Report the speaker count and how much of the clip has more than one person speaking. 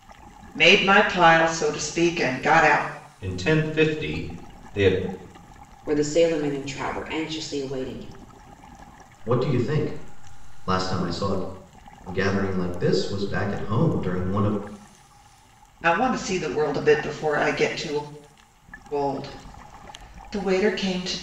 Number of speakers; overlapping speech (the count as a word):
four, no overlap